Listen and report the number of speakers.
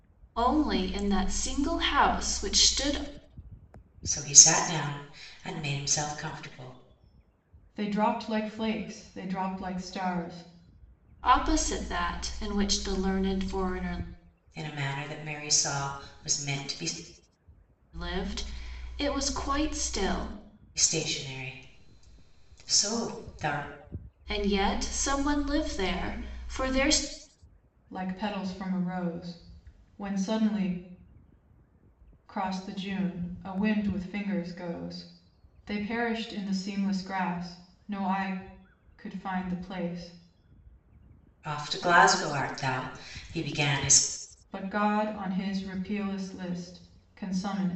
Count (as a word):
three